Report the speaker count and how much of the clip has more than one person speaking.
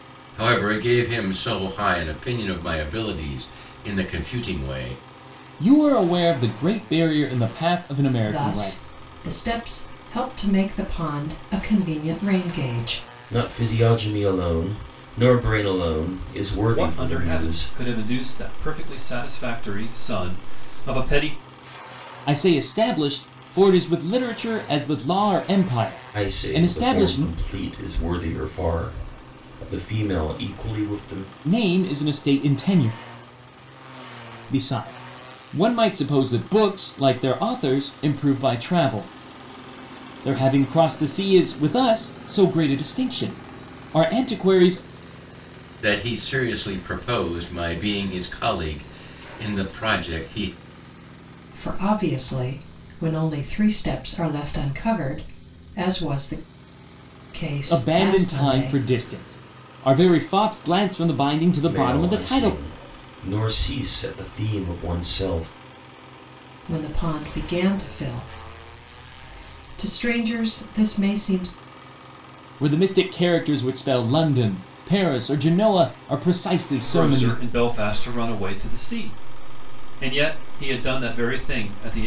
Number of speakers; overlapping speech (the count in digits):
5, about 7%